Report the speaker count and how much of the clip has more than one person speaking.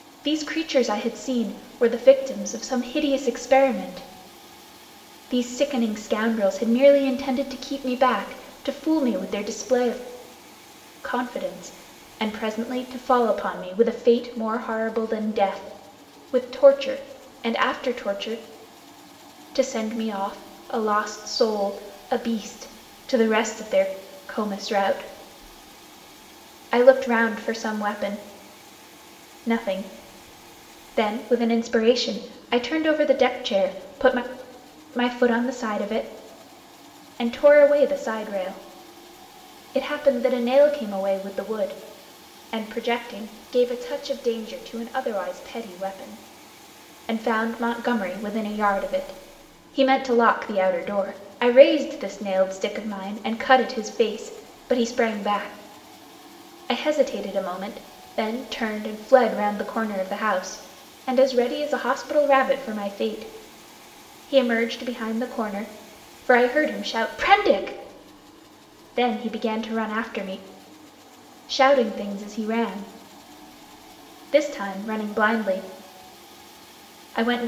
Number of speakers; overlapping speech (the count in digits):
1, no overlap